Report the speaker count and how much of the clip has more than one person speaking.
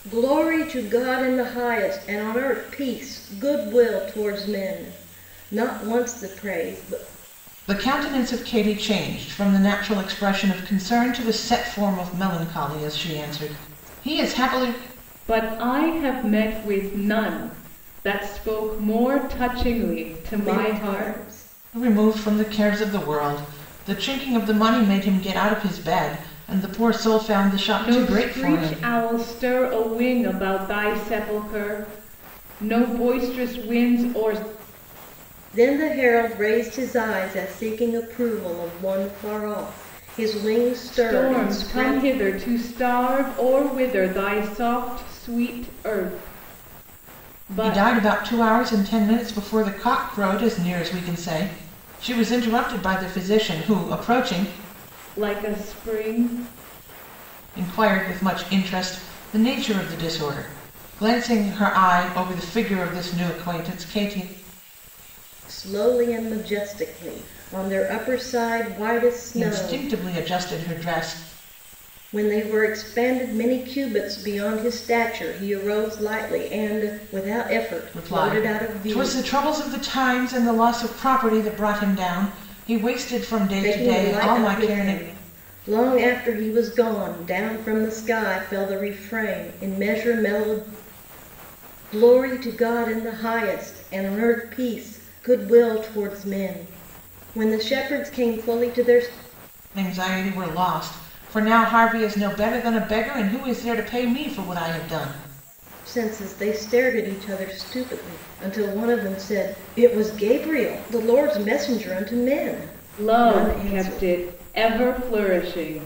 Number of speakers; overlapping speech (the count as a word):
three, about 7%